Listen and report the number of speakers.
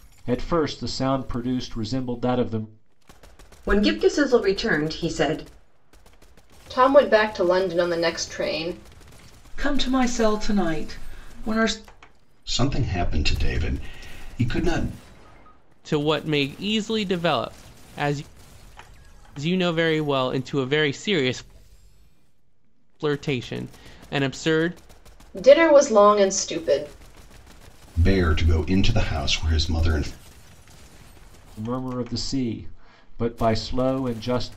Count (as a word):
six